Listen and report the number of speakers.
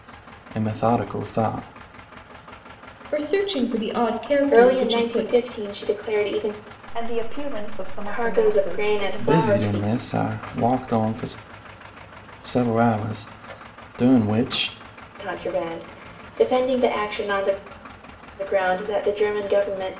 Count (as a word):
four